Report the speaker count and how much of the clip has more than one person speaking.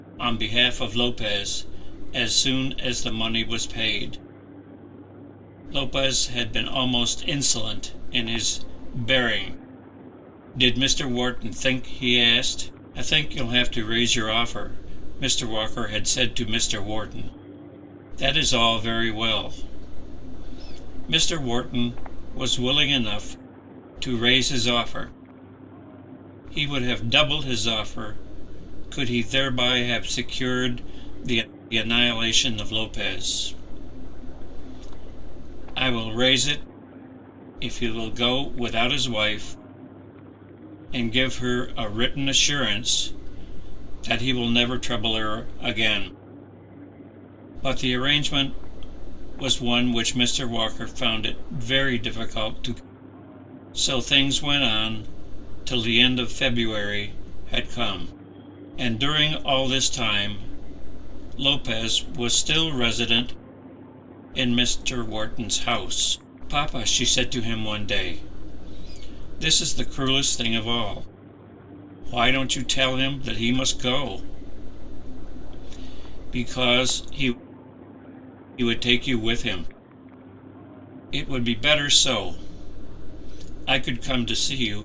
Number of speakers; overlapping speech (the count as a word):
one, no overlap